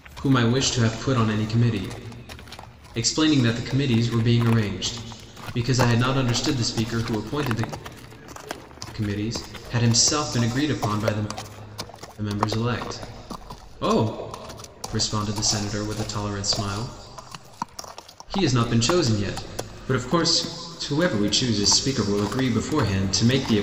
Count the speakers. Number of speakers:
1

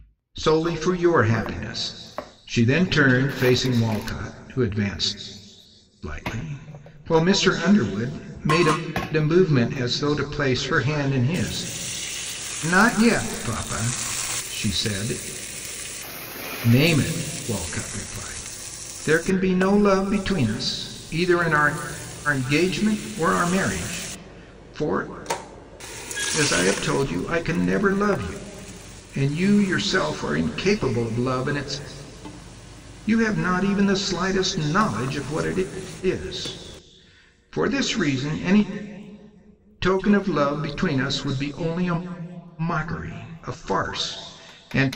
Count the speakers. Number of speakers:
1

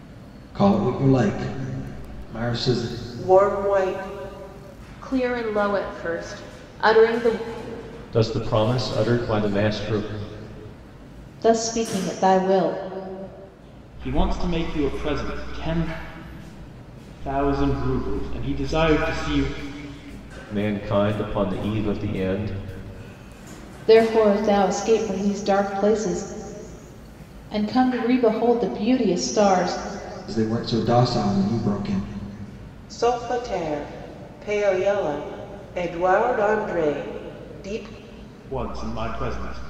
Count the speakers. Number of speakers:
6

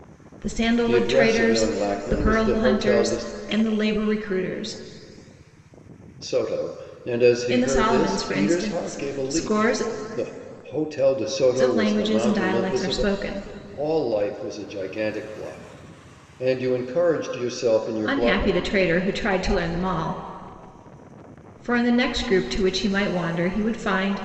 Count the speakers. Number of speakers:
2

